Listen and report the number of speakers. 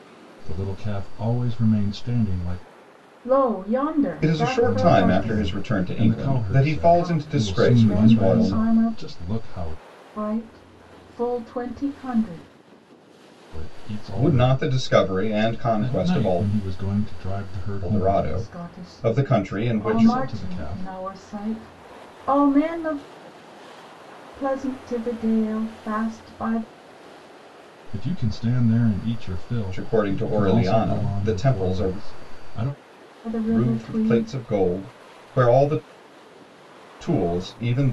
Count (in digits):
3